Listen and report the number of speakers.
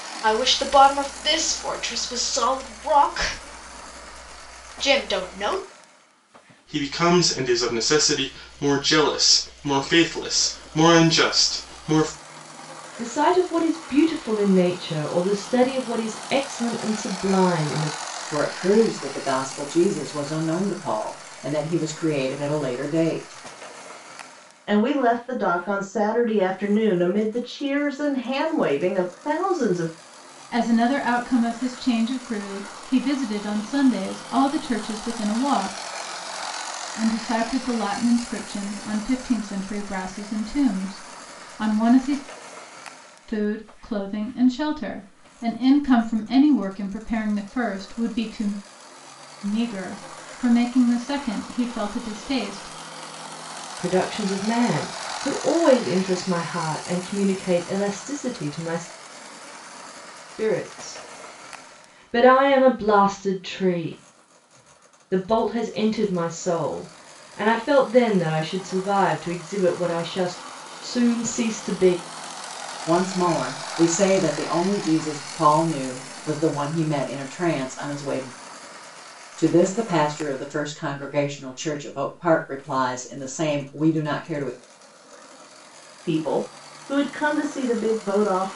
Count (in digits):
6